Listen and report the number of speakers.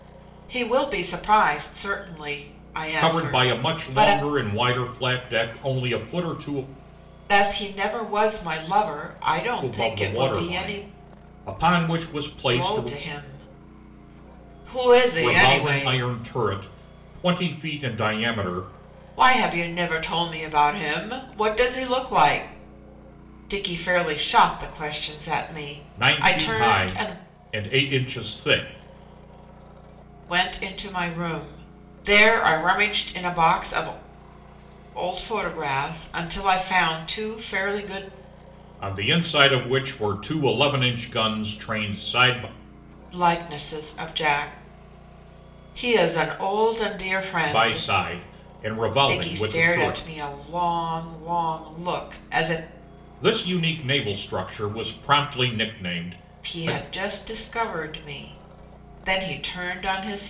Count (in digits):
2